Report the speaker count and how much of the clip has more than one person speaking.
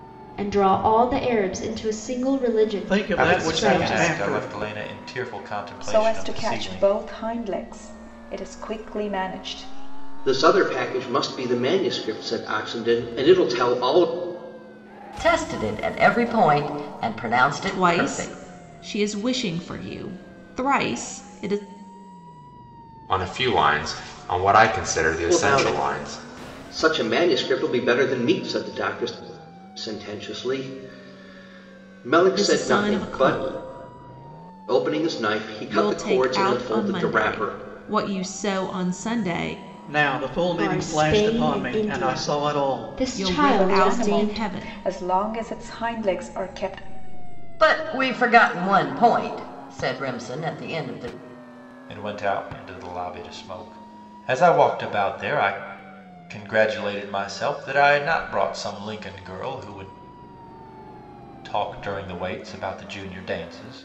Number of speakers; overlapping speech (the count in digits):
8, about 18%